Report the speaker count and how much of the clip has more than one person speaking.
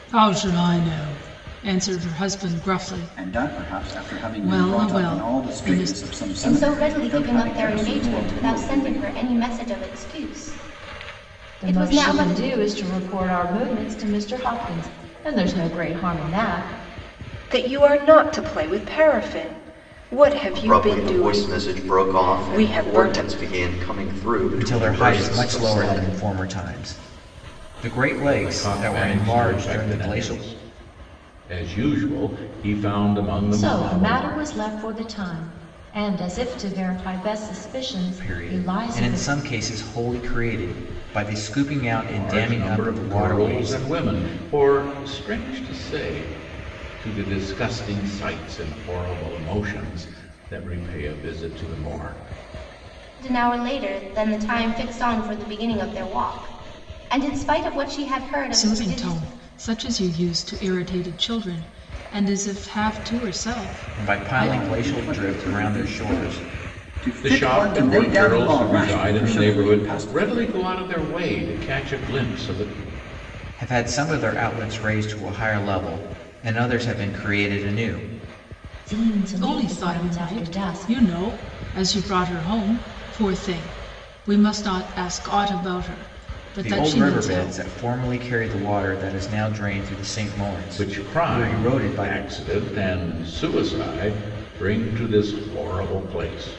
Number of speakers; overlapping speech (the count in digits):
8, about 28%